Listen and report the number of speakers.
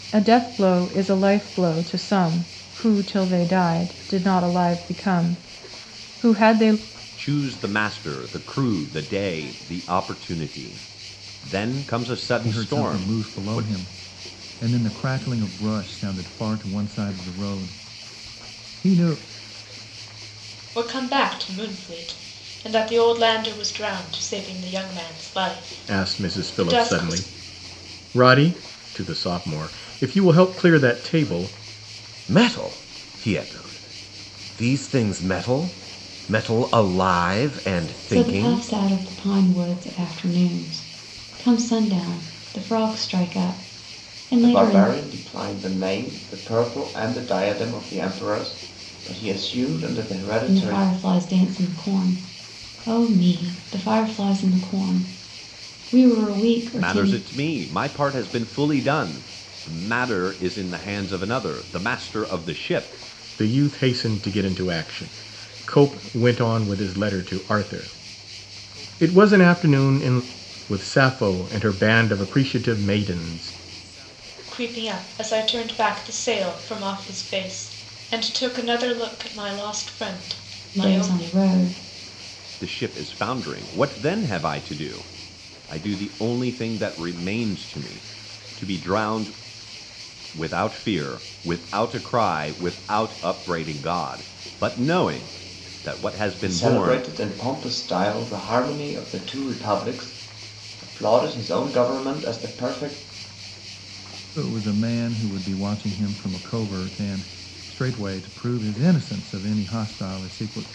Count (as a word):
eight